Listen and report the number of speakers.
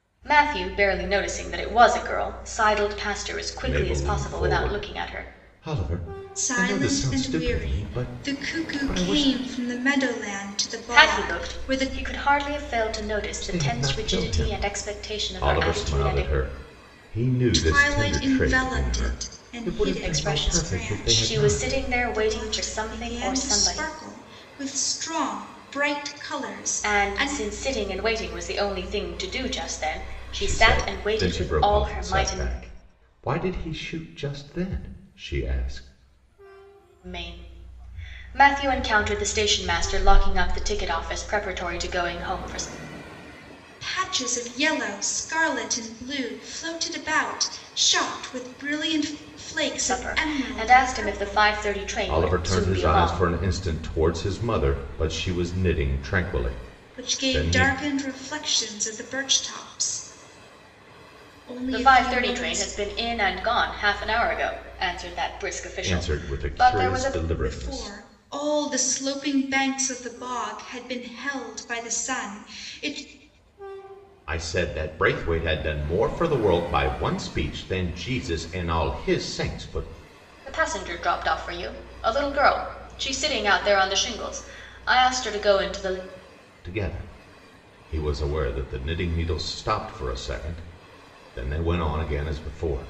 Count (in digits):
3